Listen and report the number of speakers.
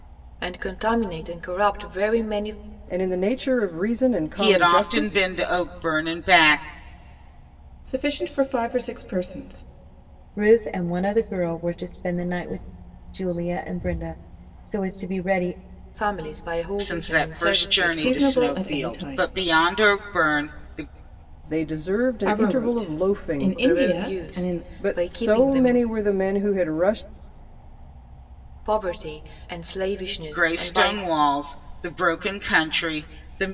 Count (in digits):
5